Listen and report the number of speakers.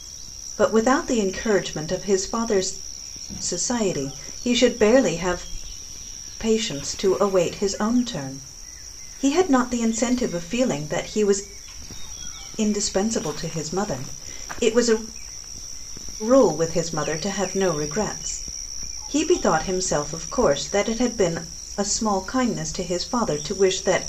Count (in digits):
1